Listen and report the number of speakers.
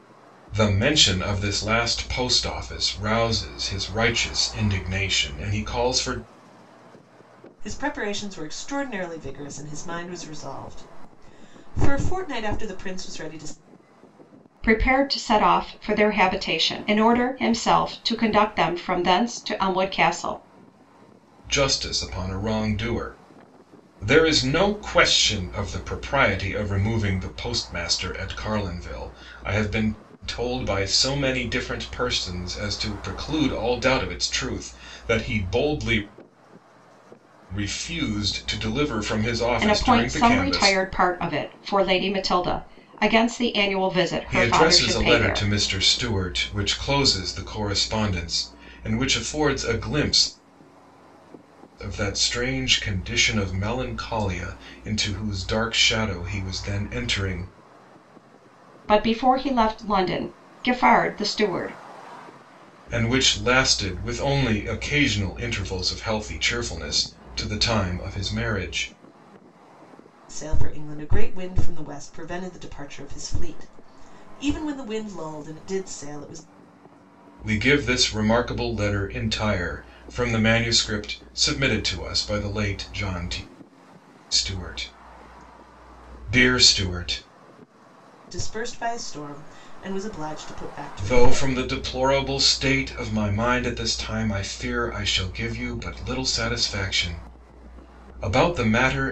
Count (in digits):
3